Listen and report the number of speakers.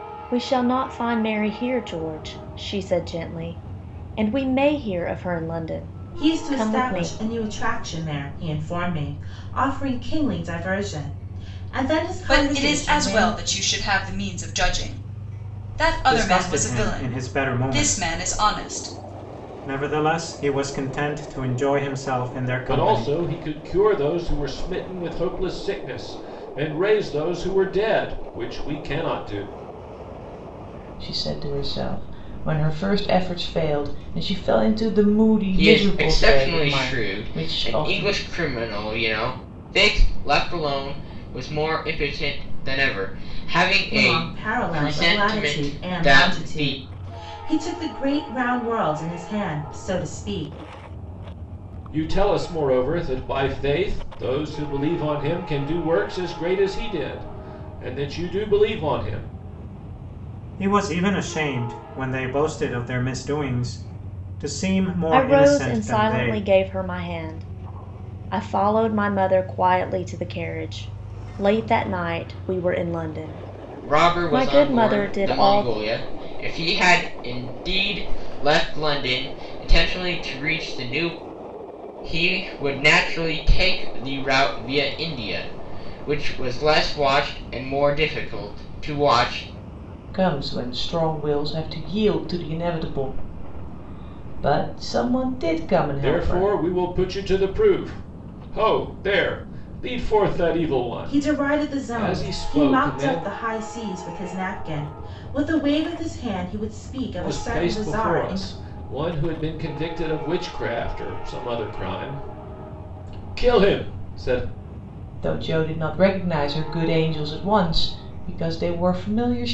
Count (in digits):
7